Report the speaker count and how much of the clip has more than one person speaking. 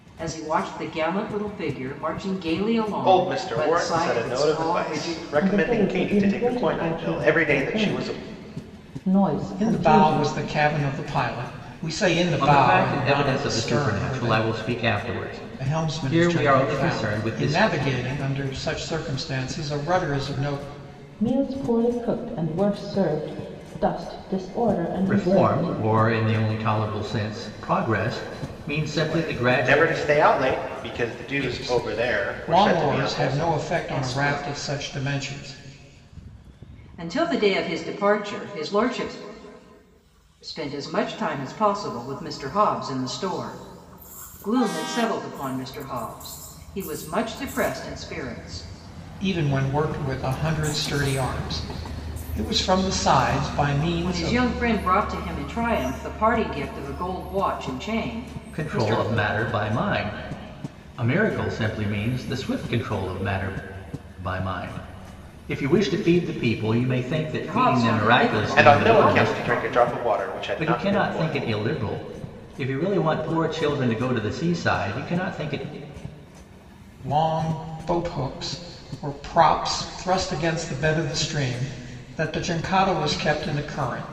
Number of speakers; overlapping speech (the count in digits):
5, about 24%